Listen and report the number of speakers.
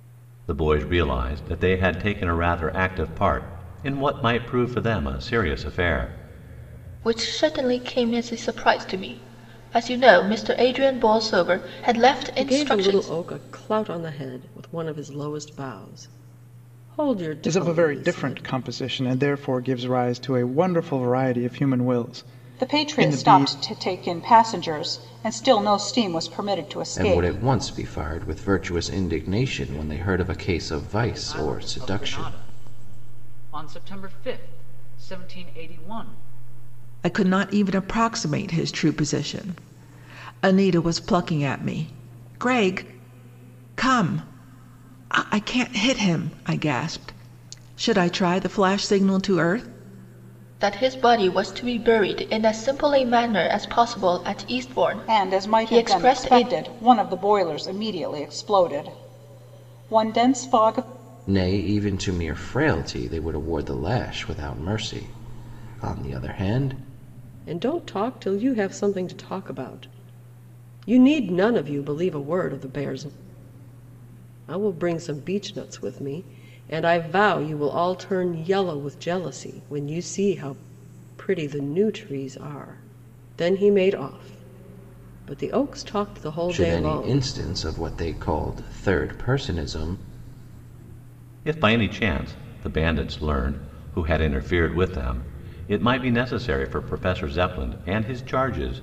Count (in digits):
8